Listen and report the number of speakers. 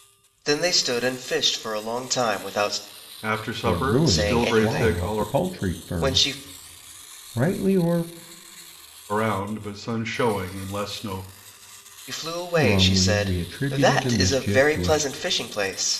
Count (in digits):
3